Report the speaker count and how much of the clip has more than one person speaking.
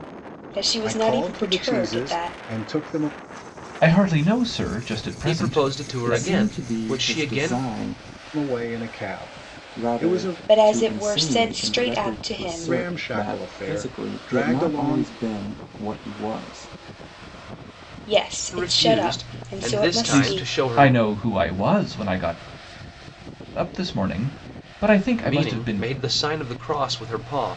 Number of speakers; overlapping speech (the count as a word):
five, about 45%